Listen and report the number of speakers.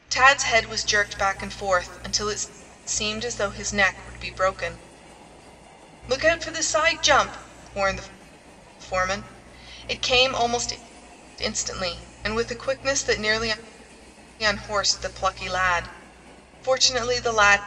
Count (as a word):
one